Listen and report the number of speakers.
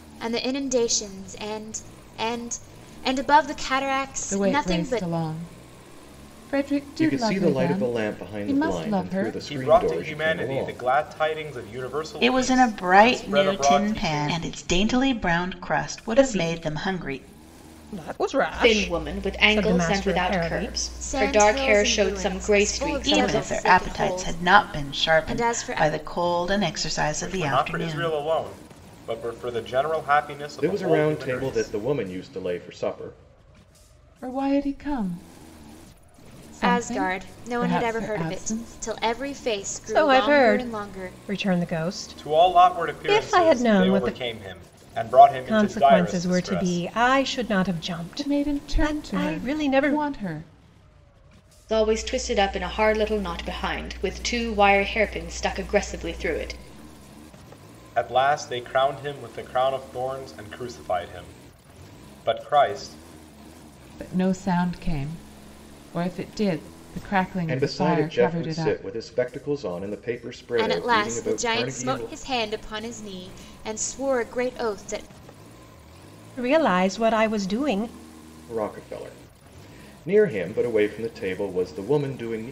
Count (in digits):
7